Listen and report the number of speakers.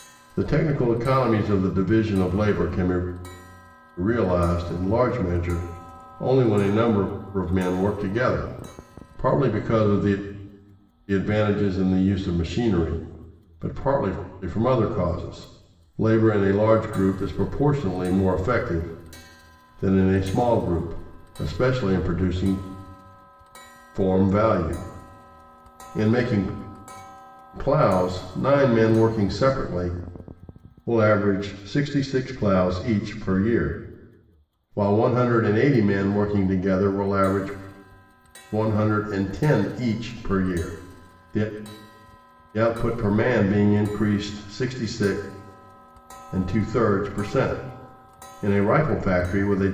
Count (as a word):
one